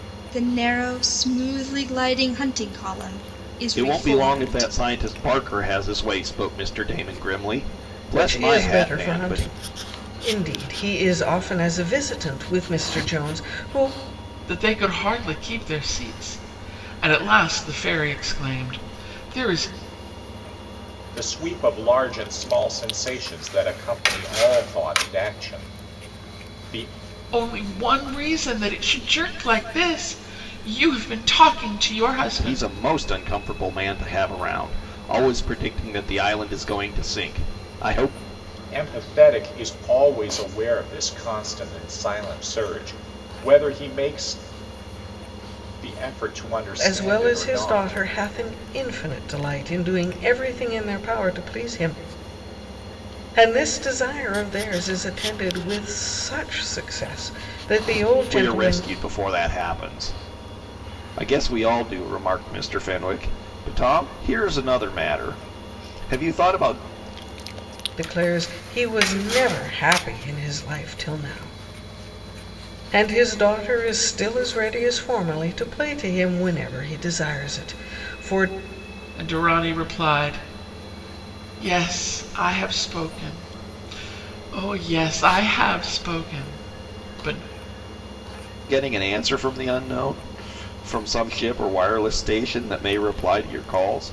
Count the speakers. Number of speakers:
five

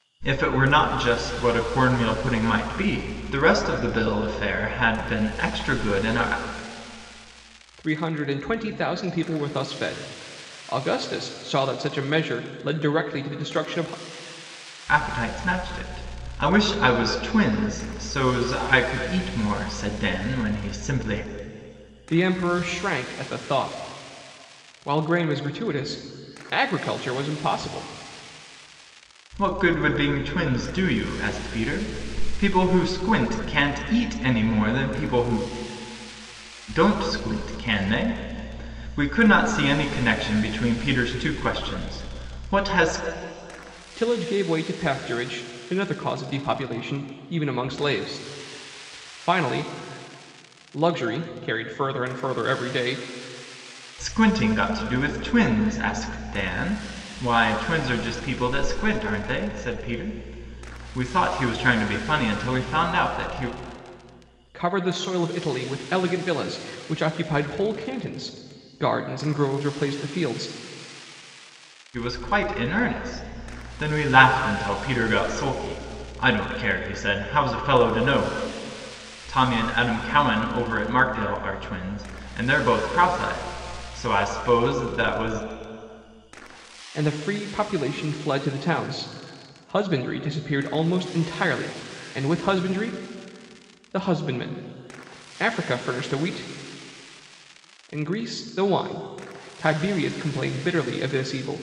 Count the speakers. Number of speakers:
two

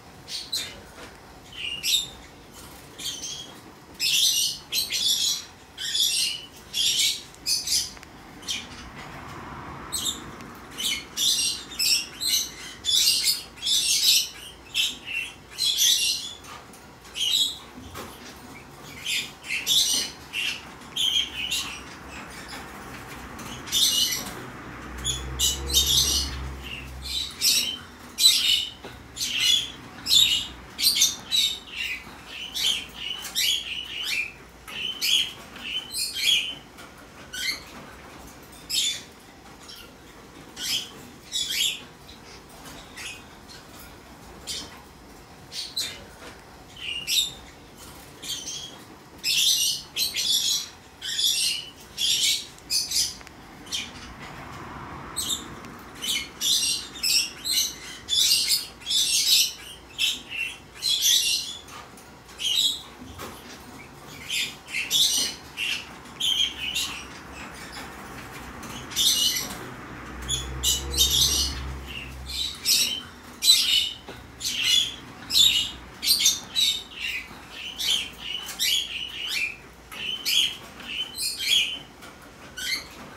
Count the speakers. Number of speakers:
zero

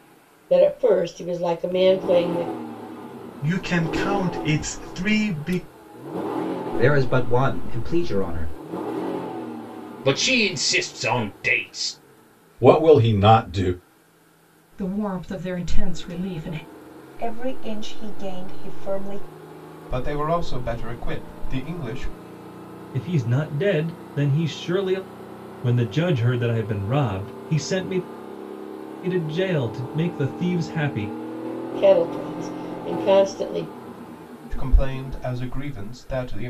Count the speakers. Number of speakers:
nine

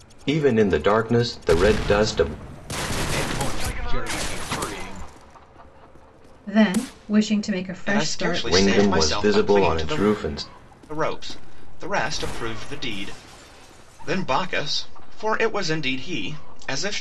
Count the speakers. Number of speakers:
four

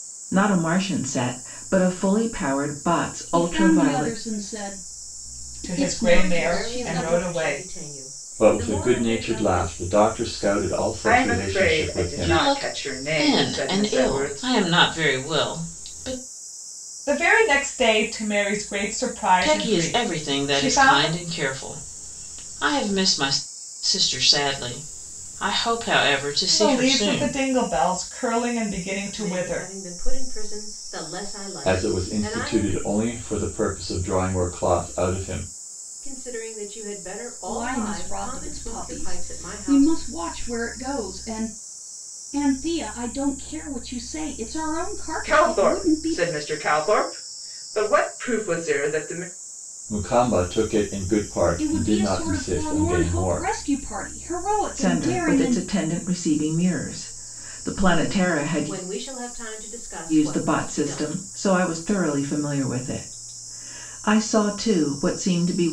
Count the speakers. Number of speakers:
seven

